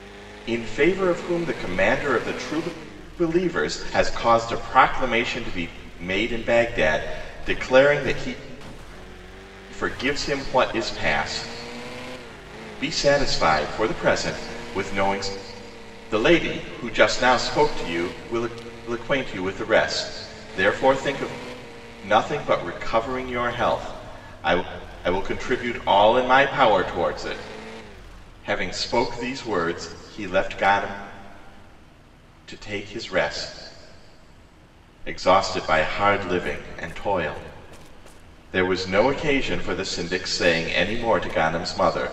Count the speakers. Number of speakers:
1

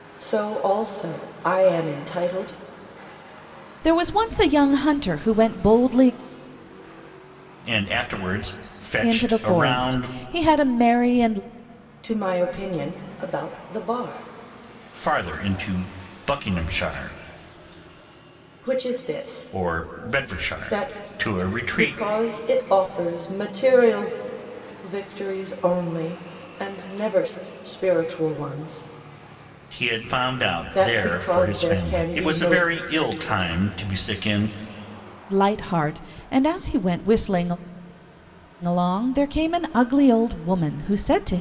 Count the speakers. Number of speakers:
3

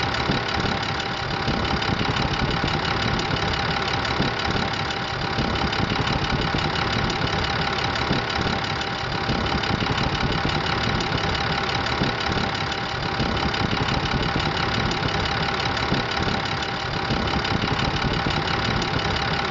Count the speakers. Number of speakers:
0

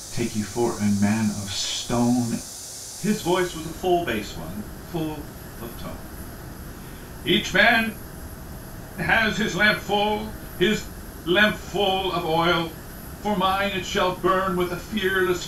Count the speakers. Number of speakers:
1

